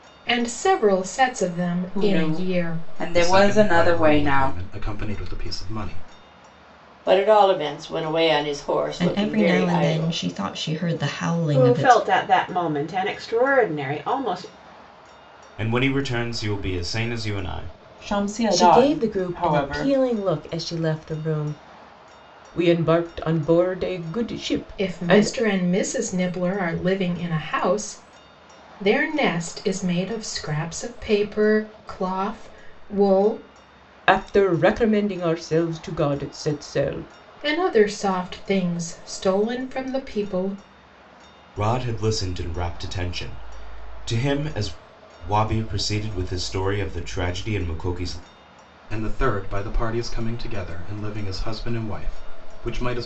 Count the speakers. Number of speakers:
nine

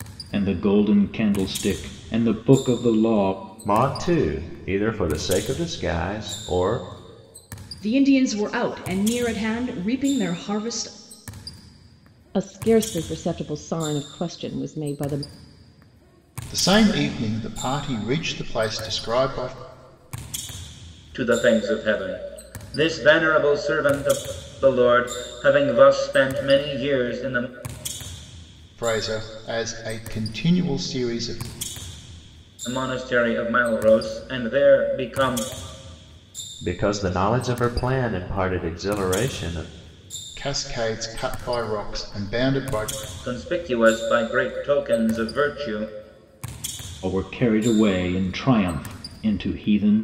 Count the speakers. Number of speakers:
six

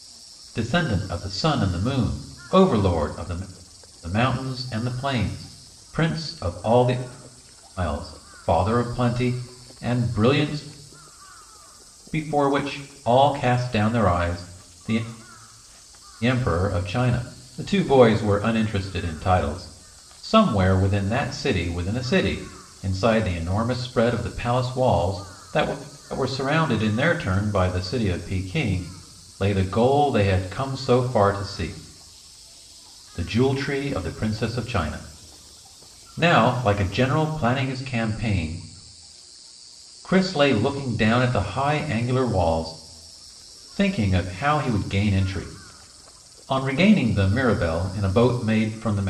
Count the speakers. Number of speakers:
one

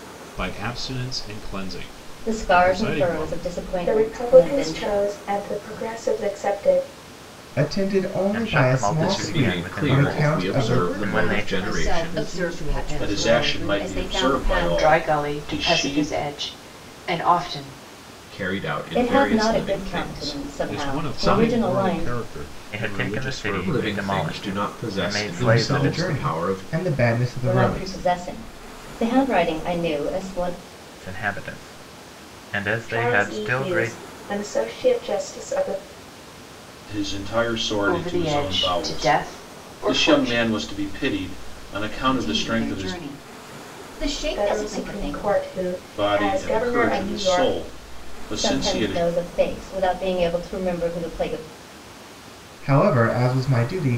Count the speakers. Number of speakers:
ten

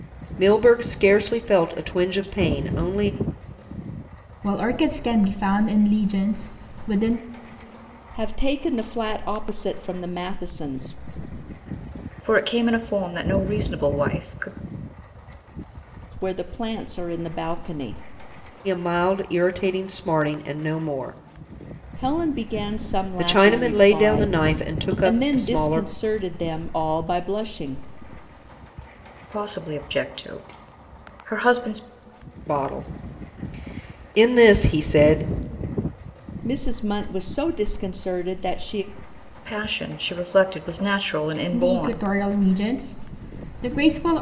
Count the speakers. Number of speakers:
four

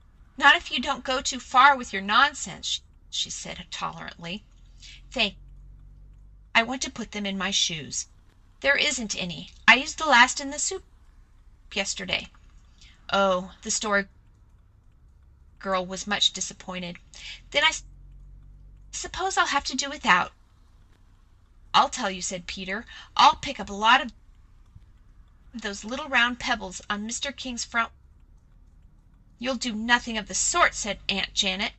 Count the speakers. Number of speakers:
one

